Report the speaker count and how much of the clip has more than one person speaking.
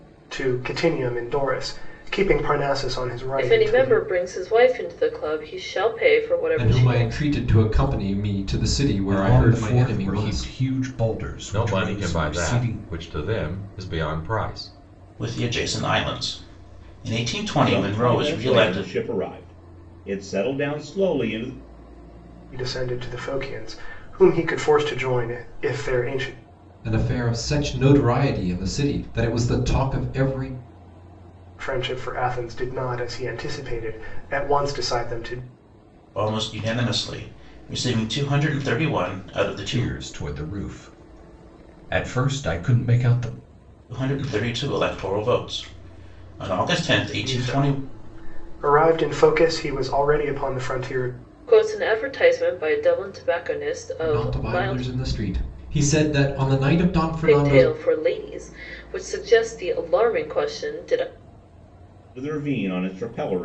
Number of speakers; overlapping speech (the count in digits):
7, about 13%